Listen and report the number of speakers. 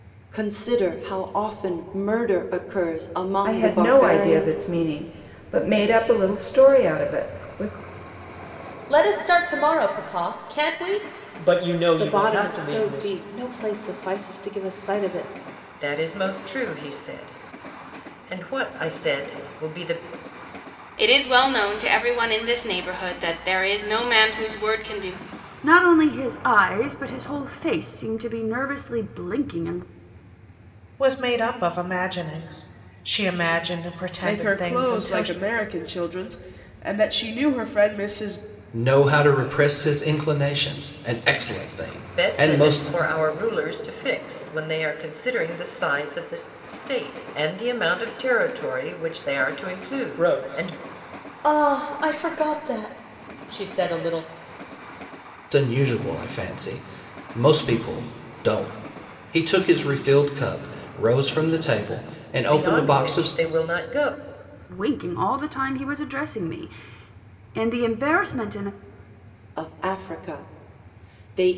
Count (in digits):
10